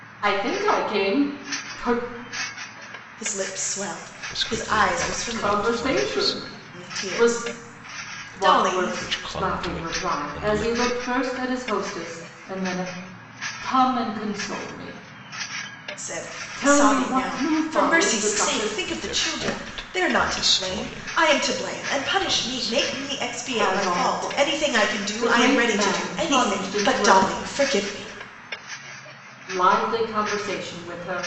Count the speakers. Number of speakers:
three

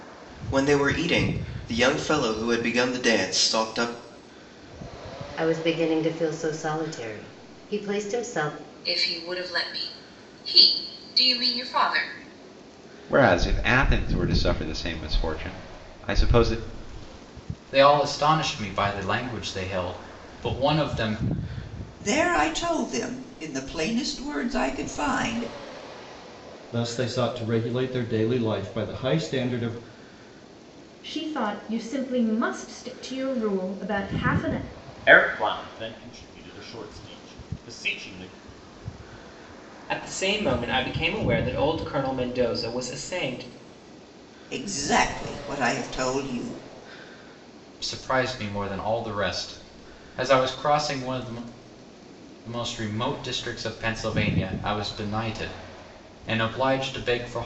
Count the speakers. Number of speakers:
ten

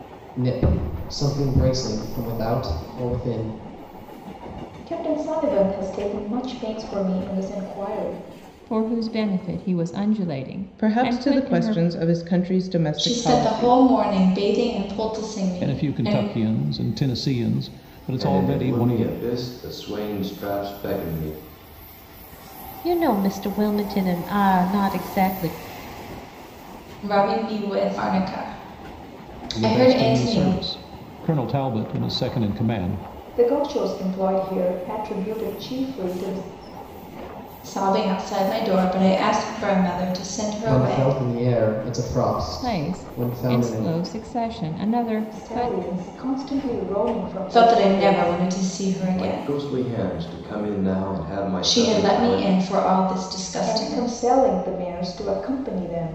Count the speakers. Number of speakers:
eight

